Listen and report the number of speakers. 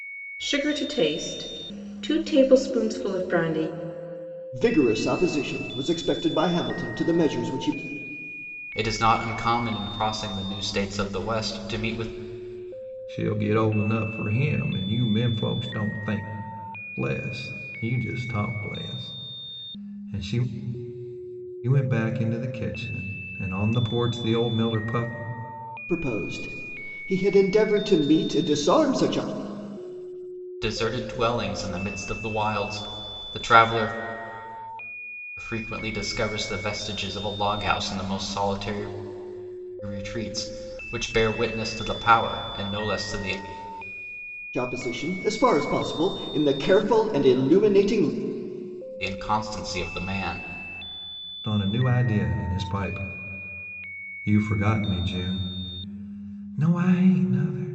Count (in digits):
4